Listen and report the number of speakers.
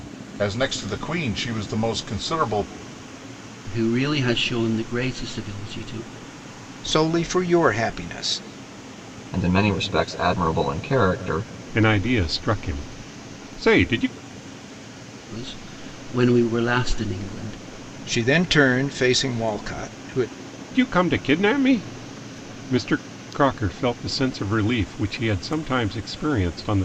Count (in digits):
5